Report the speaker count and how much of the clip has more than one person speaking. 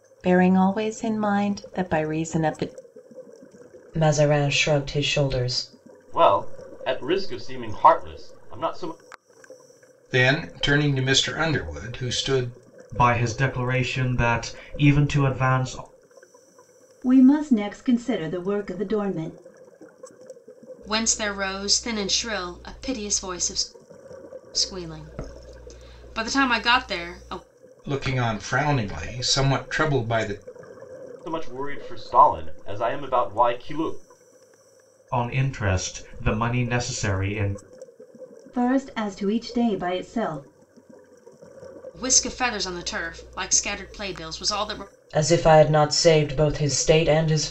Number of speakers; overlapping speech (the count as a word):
seven, no overlap